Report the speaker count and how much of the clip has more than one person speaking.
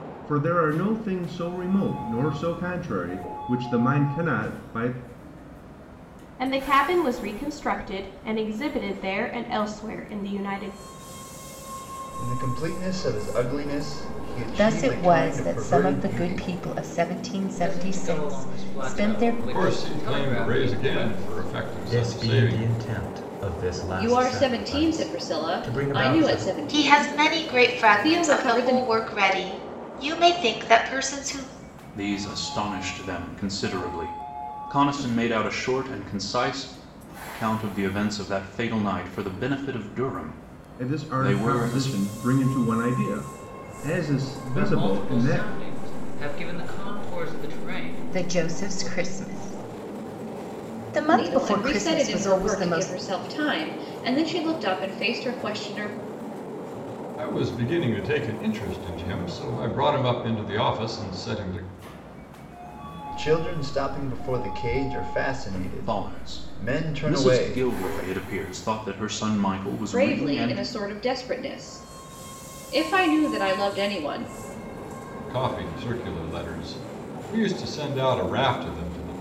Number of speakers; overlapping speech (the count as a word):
ten, about 25%